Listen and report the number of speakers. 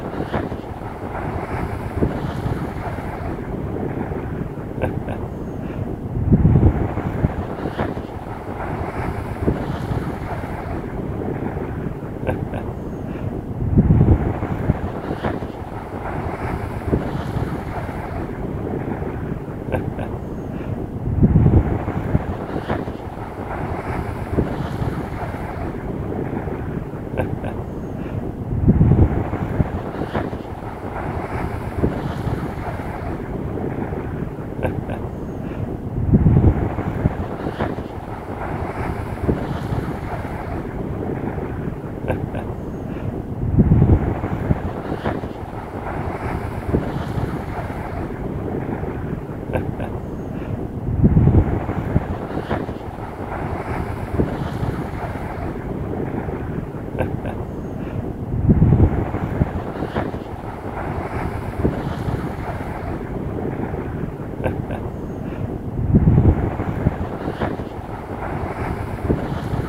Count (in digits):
0